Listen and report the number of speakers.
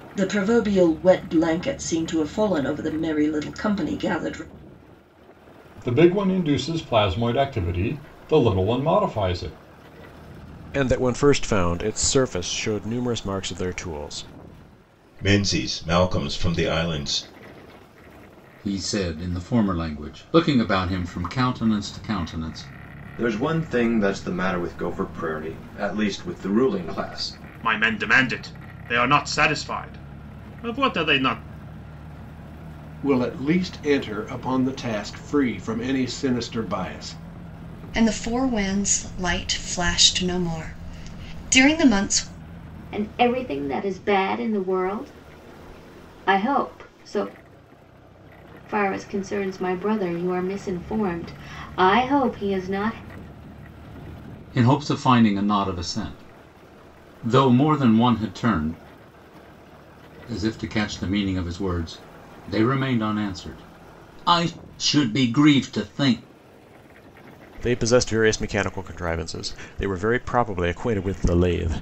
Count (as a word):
ten